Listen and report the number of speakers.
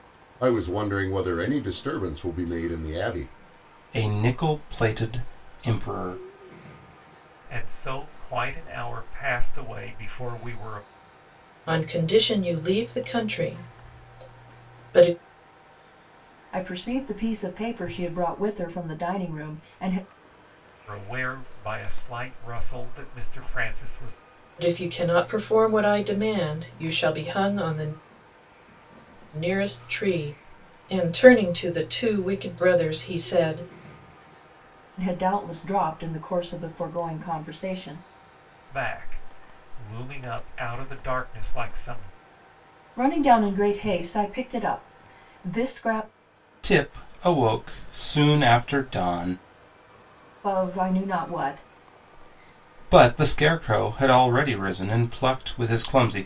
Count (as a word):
five